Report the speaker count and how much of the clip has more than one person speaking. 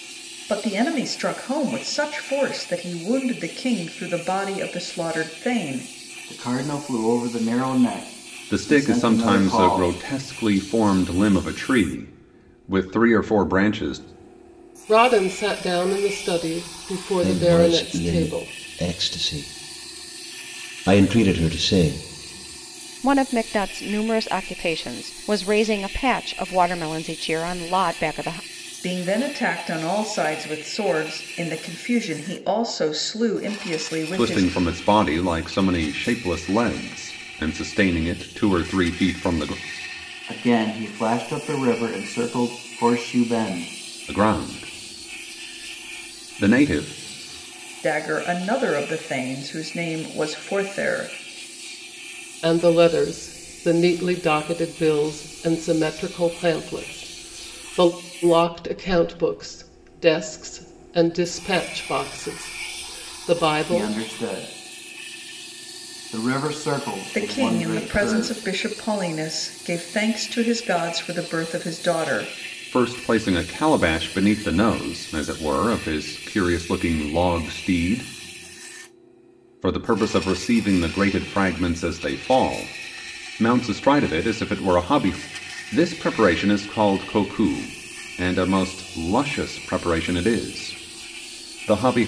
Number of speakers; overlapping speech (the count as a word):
six, about 5%